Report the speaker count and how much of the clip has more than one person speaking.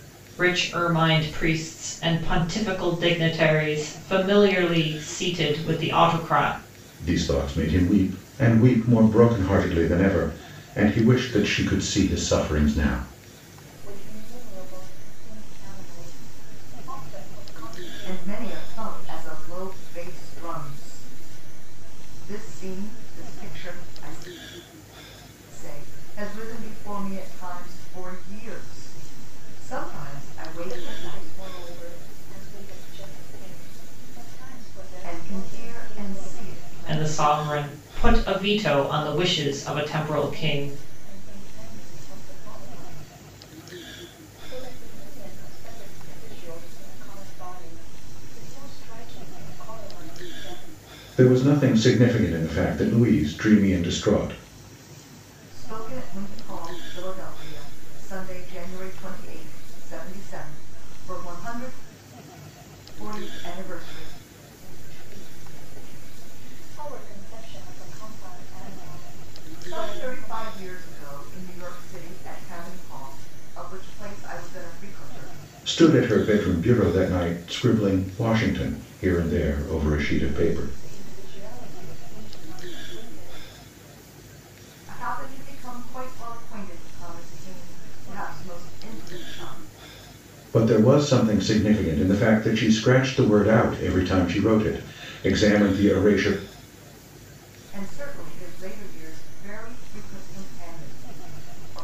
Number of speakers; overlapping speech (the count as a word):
four, about 6%